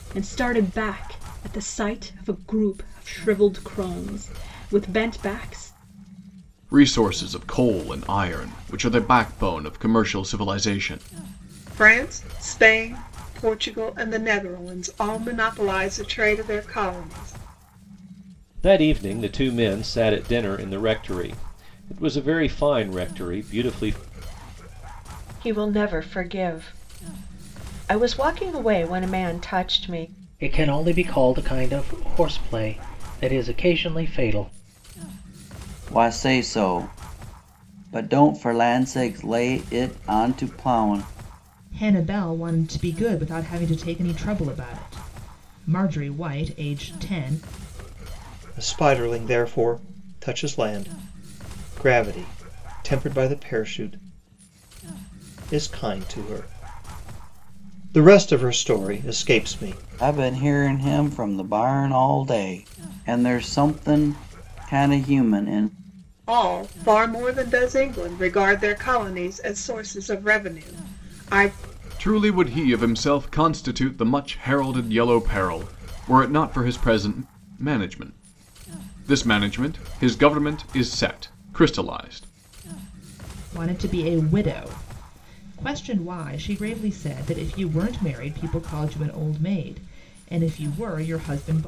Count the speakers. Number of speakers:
9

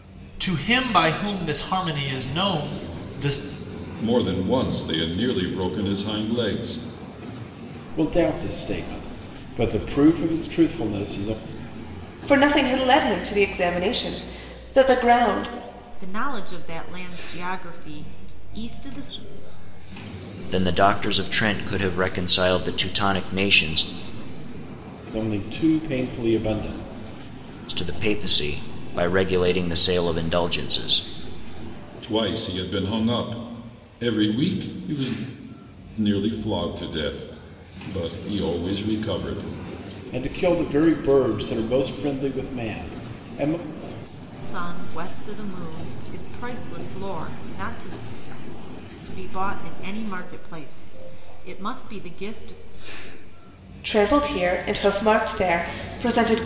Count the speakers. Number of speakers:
6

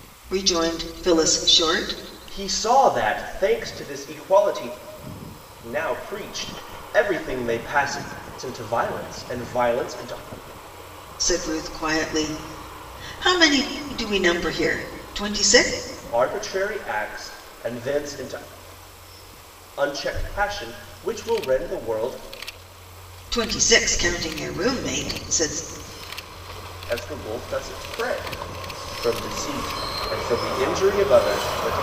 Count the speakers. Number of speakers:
2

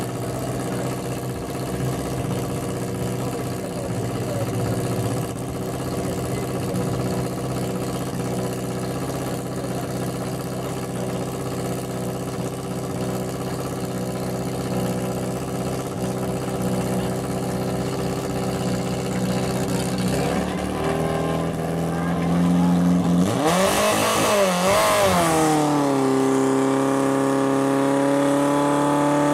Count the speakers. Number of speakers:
0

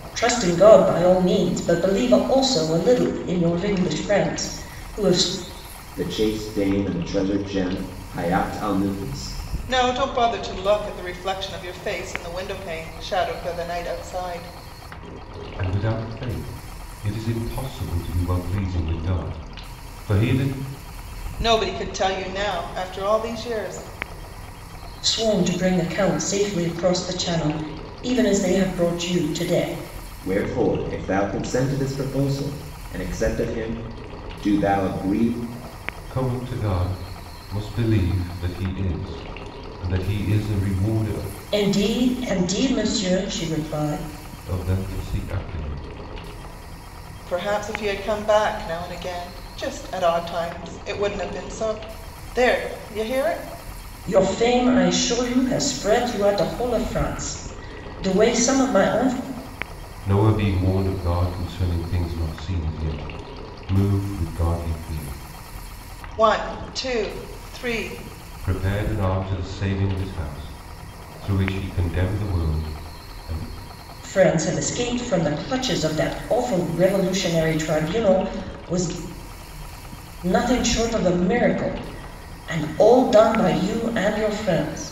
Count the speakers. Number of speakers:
4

